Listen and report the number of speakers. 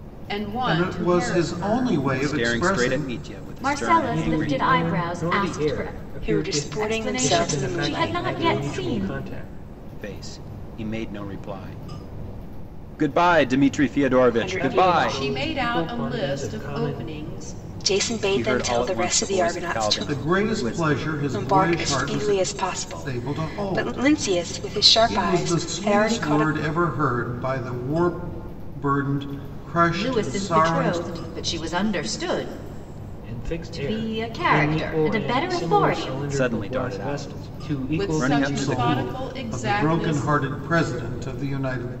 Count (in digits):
6